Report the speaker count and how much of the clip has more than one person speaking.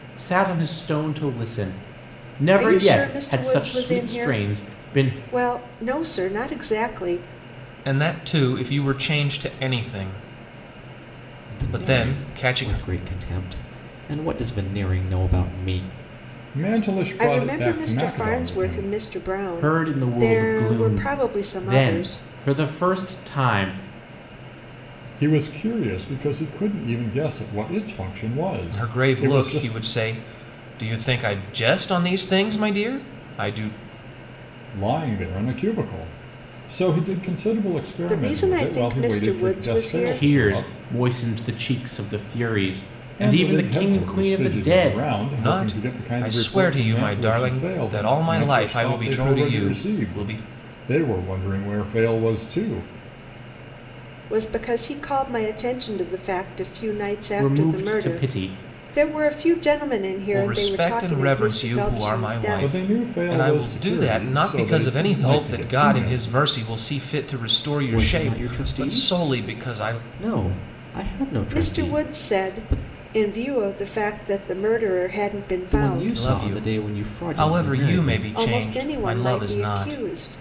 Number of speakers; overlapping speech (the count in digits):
5, about 42%